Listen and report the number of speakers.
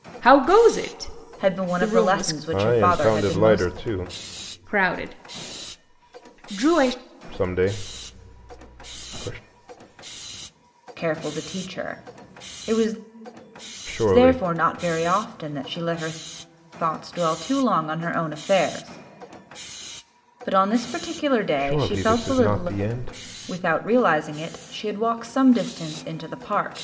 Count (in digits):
3